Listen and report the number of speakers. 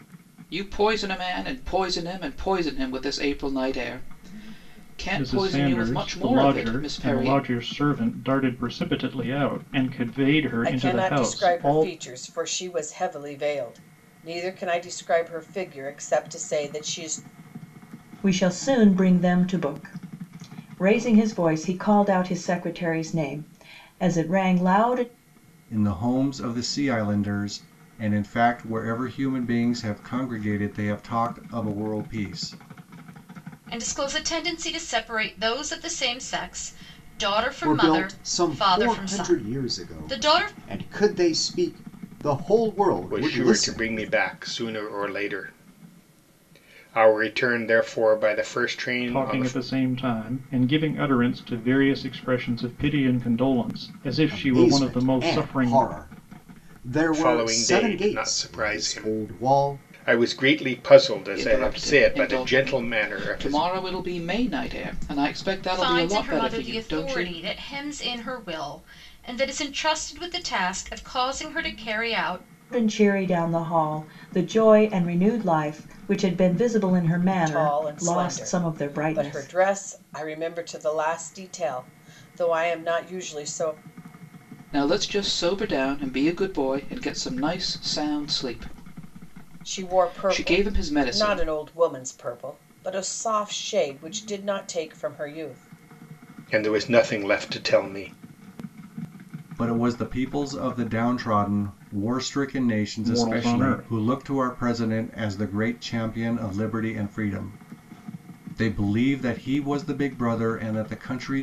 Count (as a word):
eight